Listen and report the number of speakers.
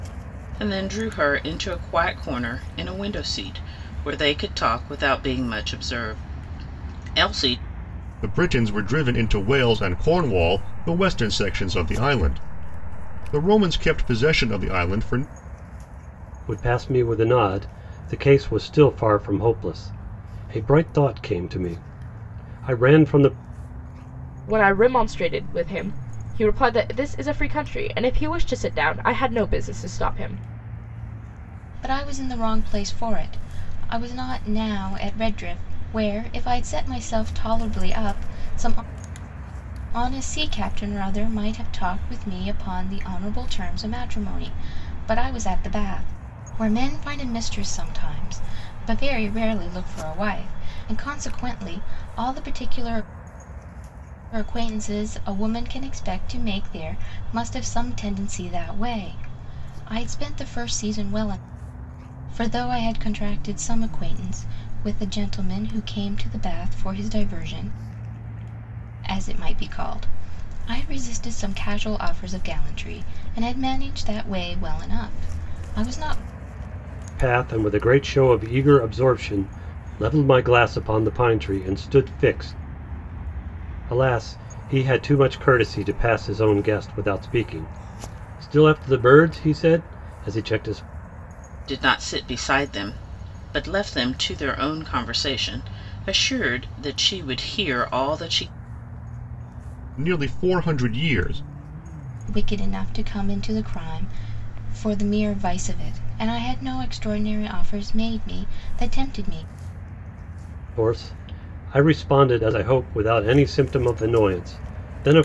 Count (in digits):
5